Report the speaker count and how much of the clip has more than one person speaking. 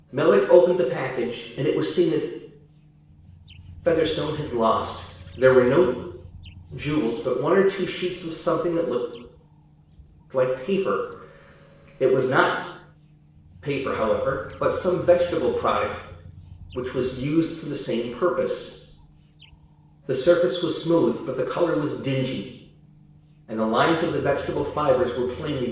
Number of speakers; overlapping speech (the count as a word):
one, no overlap